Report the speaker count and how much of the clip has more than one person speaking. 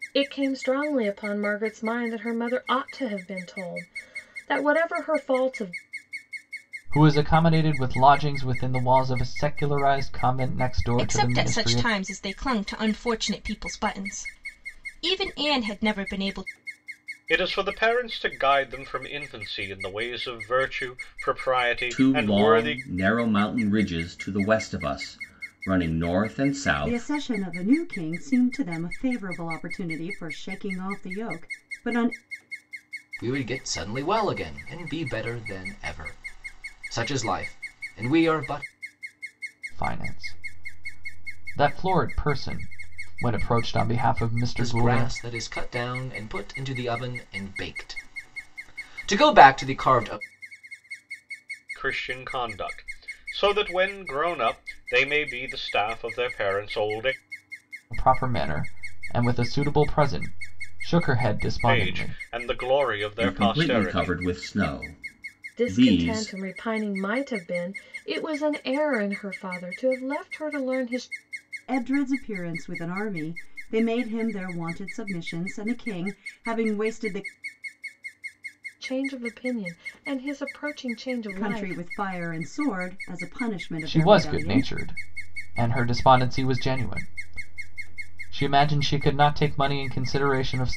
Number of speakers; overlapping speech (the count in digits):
7, about 7%